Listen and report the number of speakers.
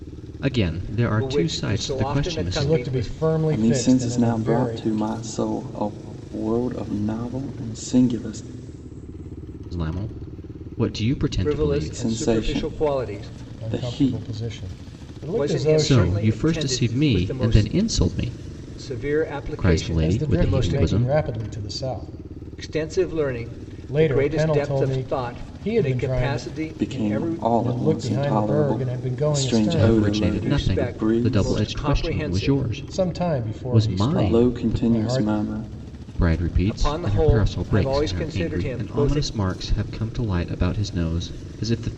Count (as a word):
four